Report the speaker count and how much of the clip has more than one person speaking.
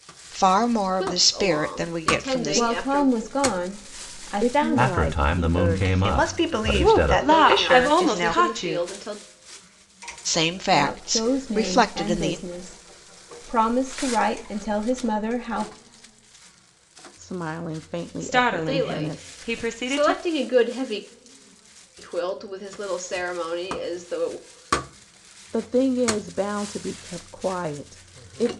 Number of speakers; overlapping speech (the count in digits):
7, about 36%